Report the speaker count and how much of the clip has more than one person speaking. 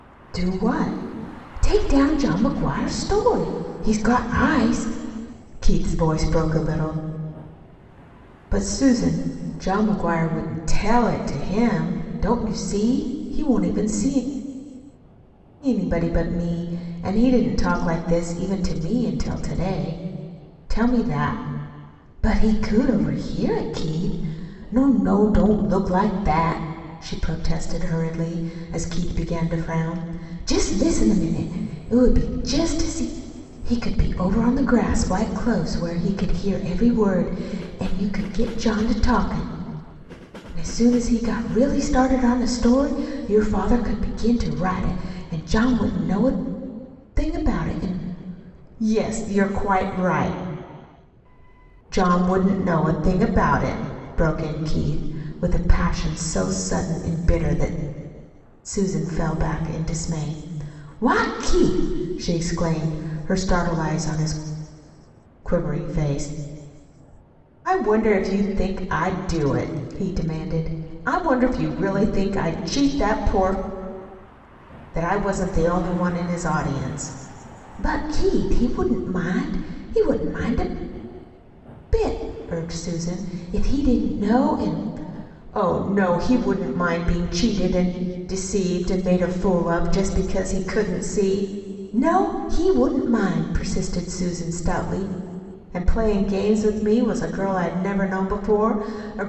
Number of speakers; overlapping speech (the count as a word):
one, no overlap